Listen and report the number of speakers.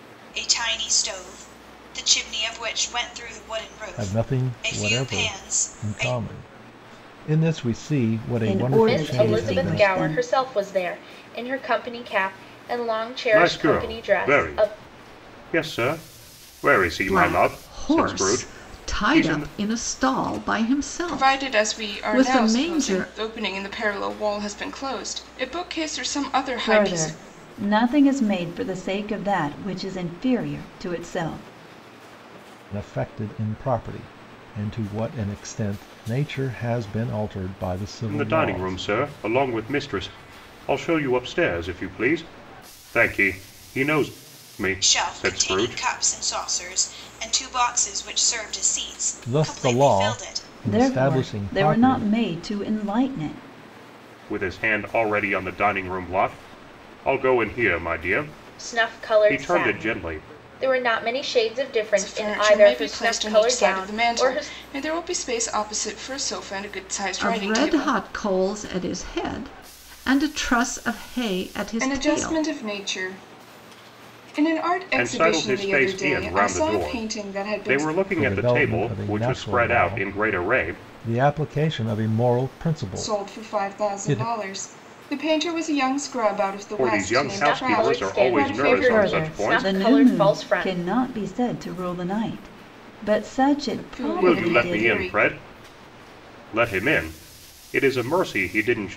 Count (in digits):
7